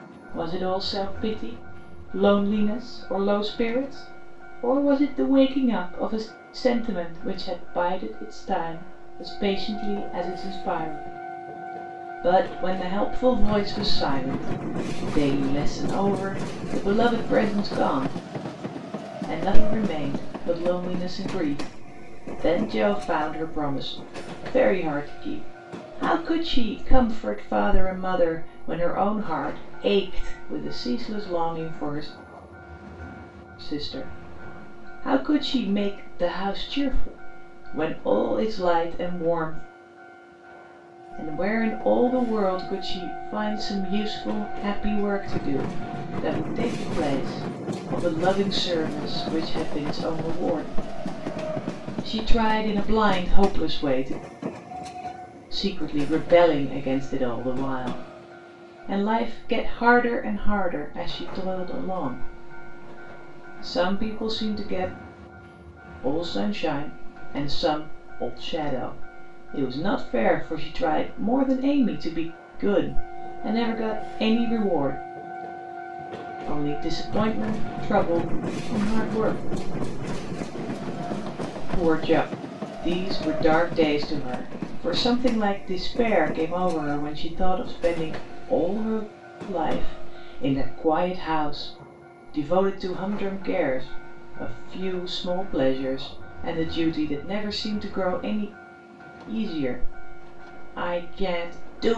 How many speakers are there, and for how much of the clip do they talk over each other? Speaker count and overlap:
one, no overlap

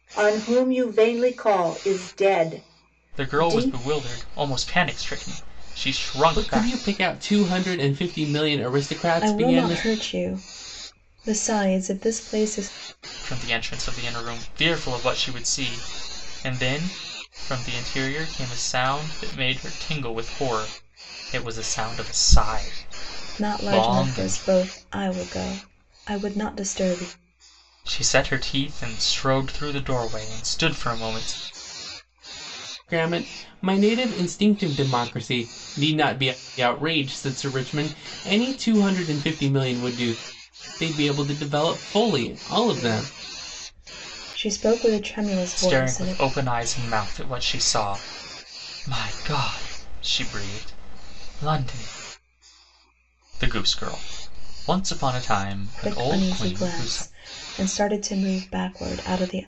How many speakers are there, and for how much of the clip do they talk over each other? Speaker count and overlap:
four, about 9%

